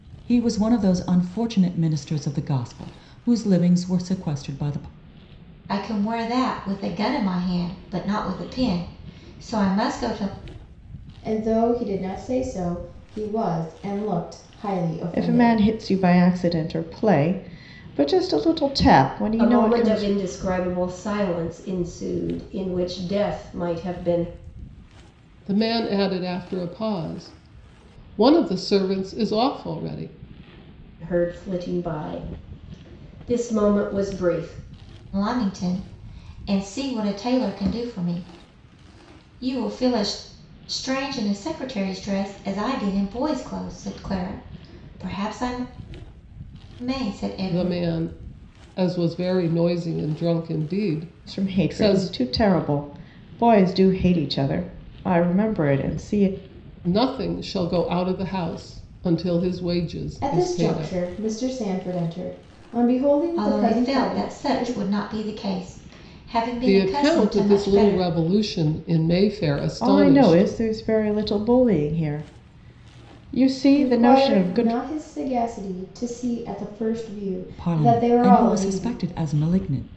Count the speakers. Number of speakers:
6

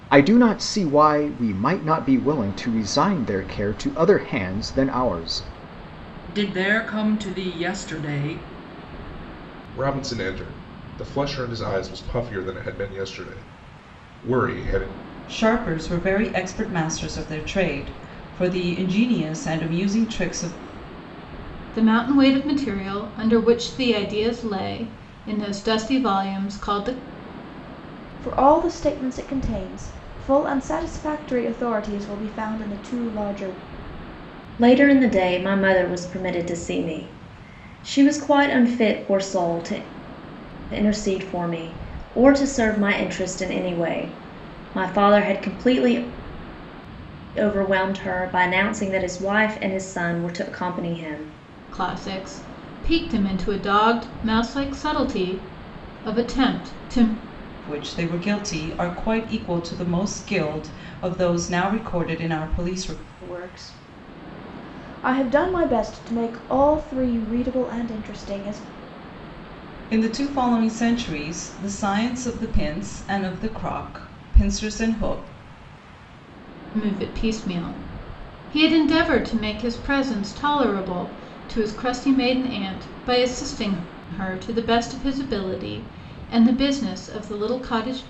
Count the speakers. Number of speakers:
7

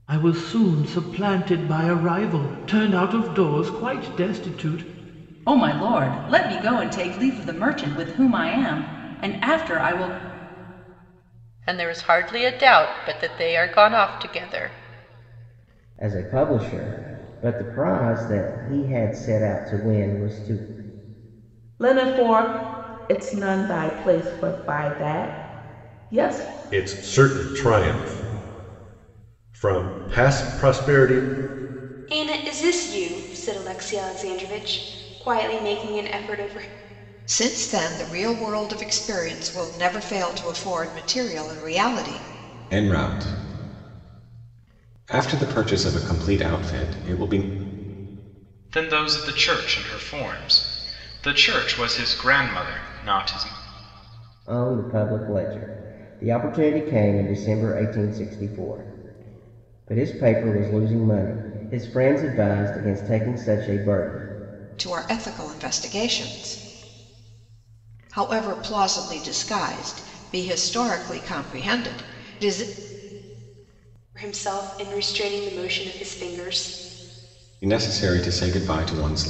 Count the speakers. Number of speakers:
10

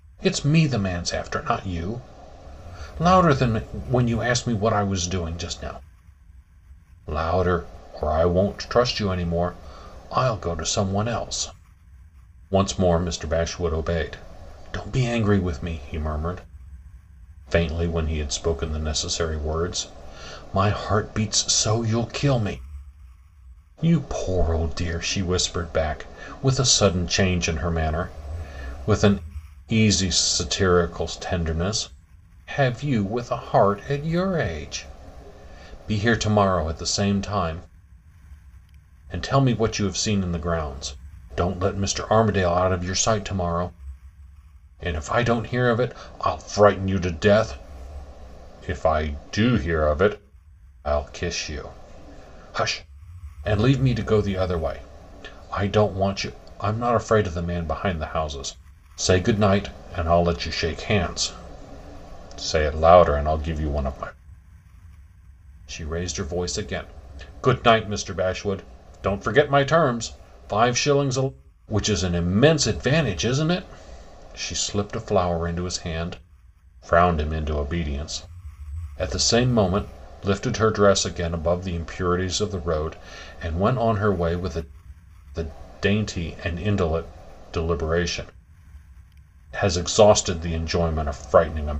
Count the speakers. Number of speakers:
1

